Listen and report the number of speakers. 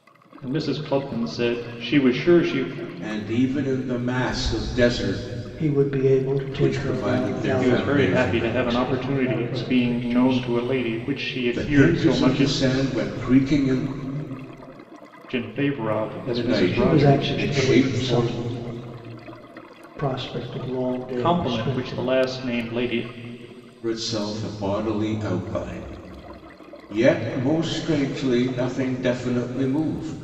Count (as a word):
three